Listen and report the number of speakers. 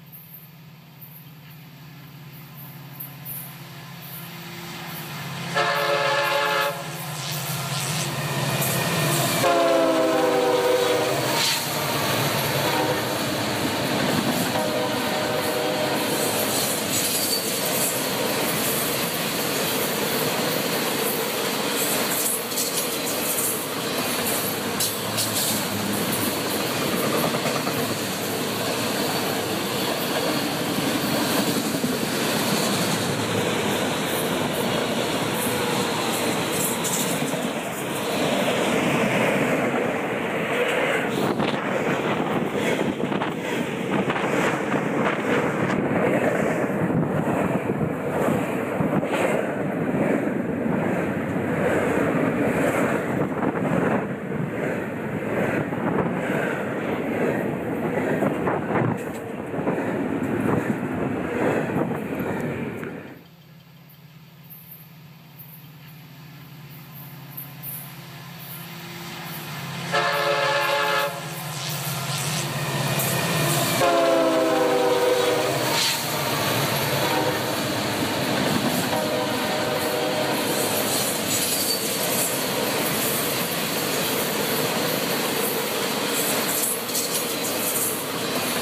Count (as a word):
zero